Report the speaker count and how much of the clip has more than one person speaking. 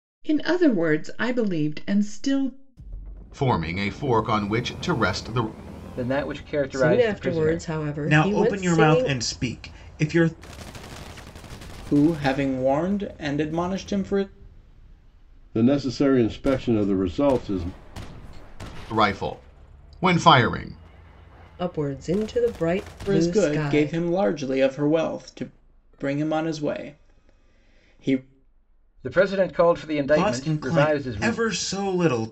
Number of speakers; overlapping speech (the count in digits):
7, about 13%